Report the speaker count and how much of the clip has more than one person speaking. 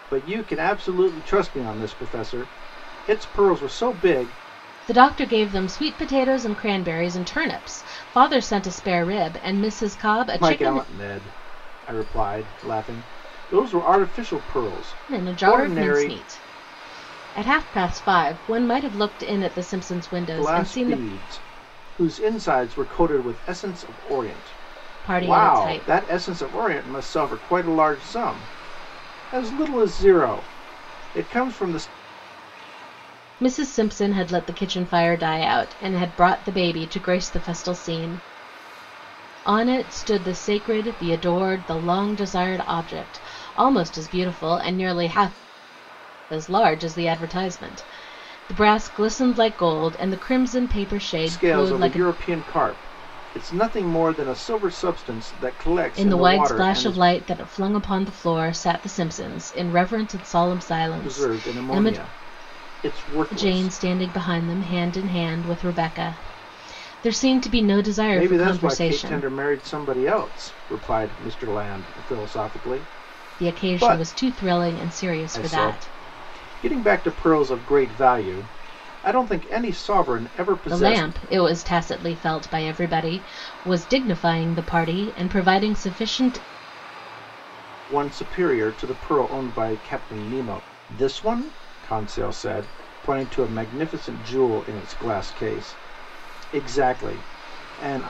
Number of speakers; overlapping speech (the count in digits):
2, about 10%